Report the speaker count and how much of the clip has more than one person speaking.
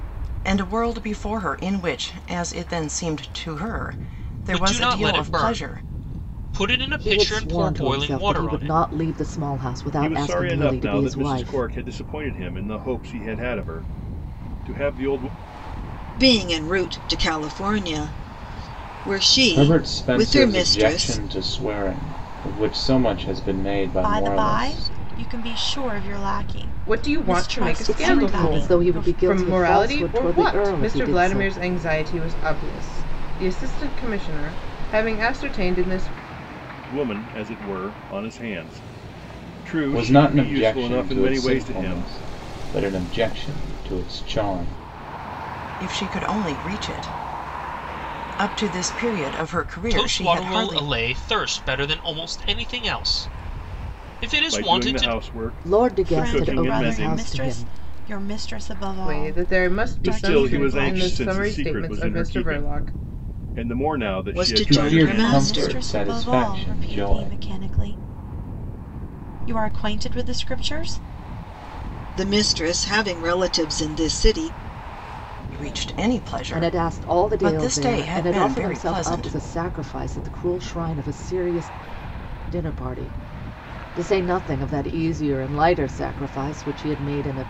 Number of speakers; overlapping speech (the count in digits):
8, about 32%